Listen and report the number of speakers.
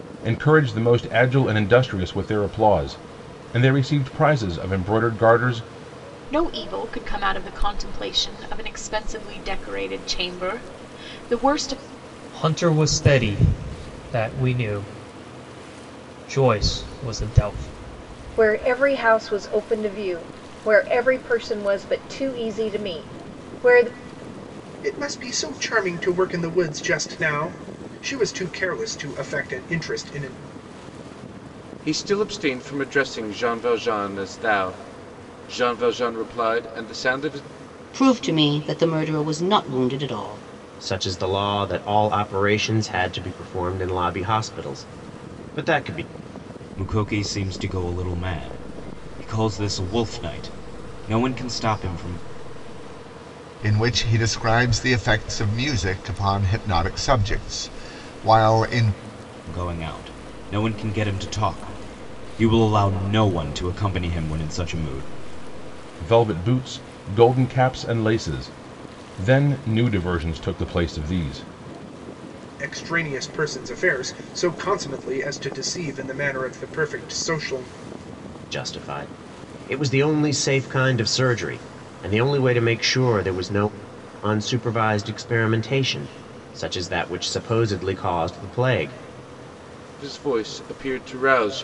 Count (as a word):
ten